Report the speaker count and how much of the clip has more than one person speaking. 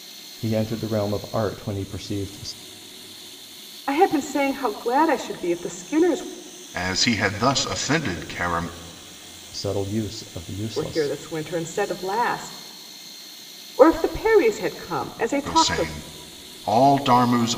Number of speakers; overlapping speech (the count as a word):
three, about 6%